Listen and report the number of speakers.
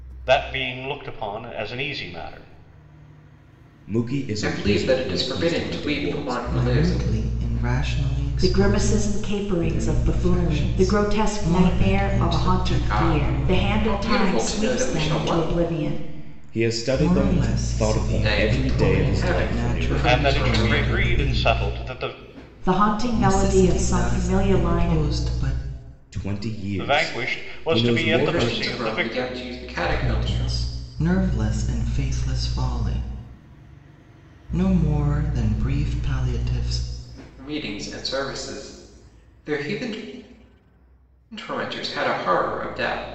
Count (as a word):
five